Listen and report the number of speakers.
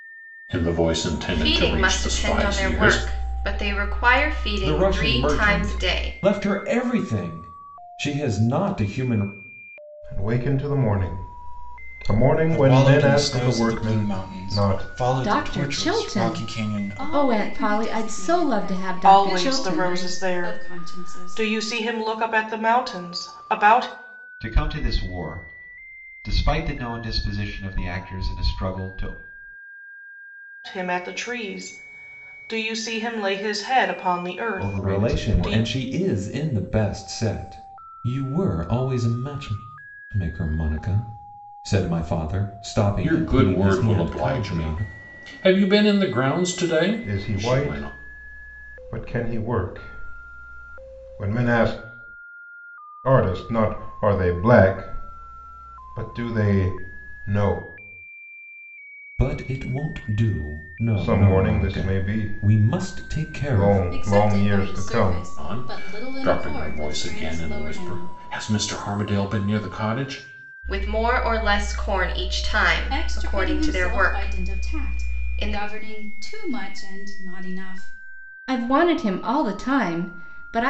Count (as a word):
nine